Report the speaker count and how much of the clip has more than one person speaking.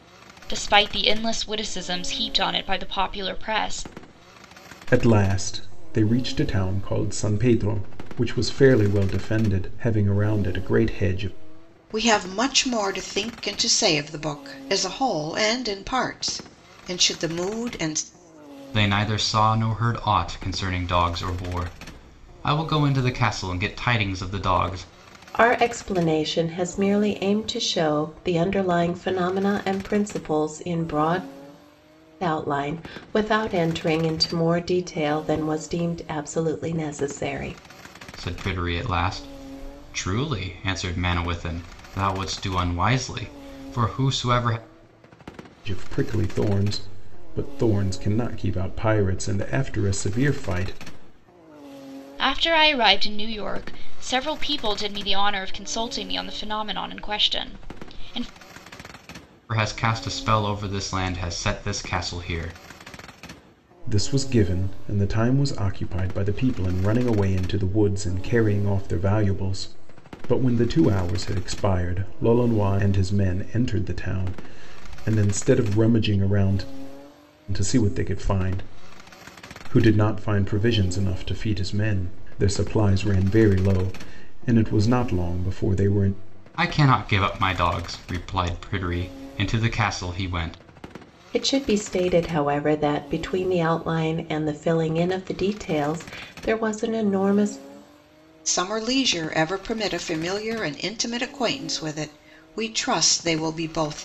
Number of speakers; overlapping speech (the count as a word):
five, no overlap